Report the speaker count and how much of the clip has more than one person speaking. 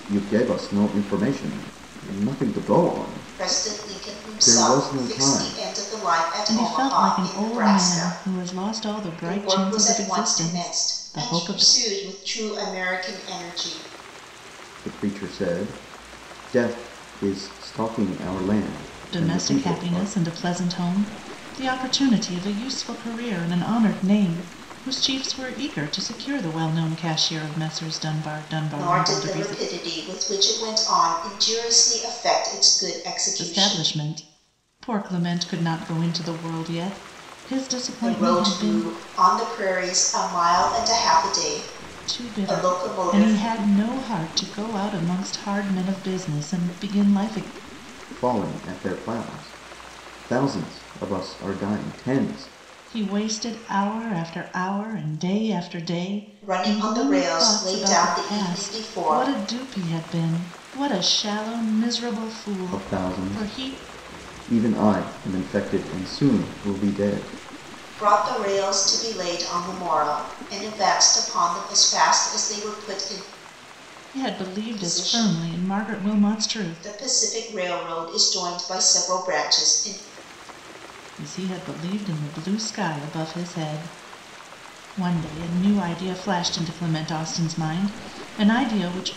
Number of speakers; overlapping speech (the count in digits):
3, about 20%